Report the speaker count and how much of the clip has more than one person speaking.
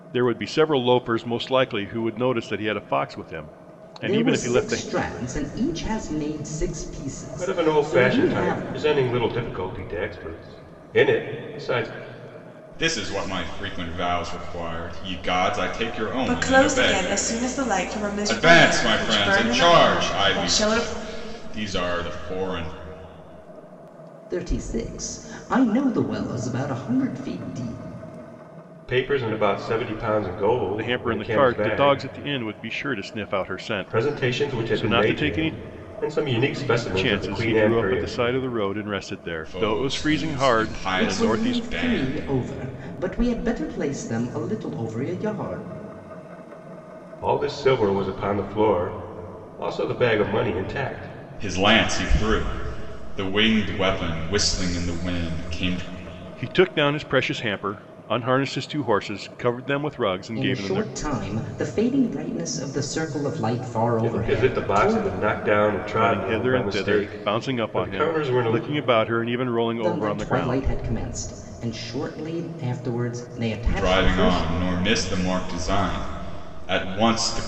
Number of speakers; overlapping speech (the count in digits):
5, about 25%